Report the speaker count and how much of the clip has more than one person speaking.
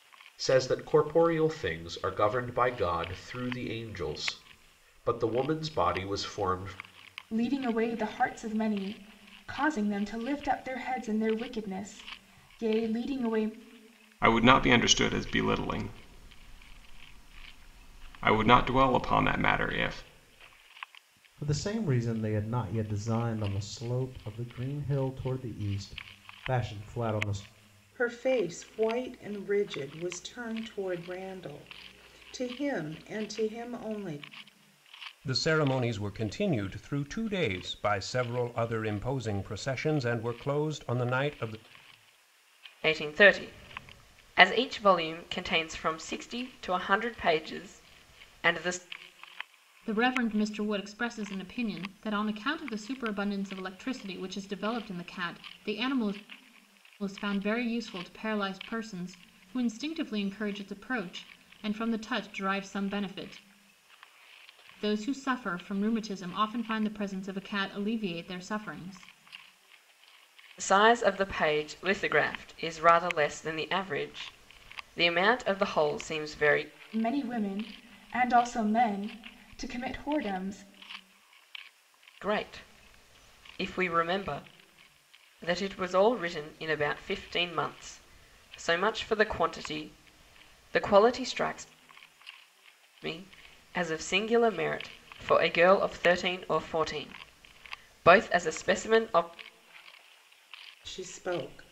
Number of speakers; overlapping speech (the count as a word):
eight, no overlap